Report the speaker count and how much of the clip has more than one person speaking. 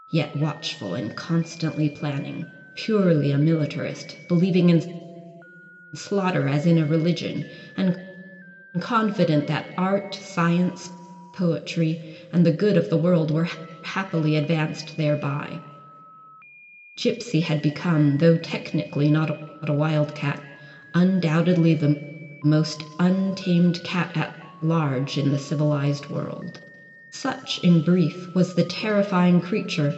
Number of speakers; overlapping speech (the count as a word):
one, no overlap